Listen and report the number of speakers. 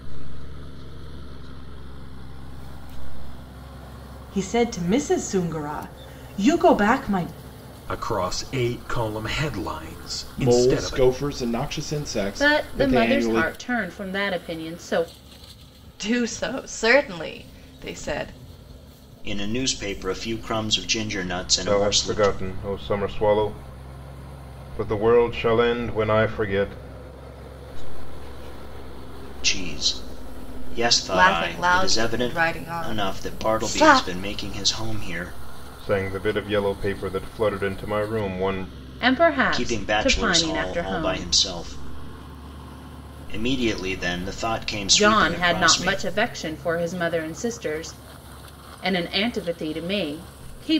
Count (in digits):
8